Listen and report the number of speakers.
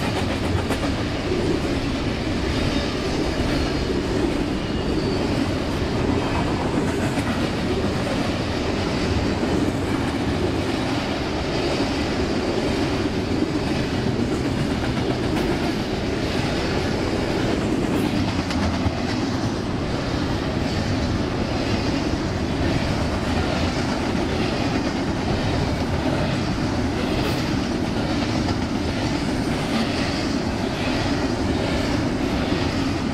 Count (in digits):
0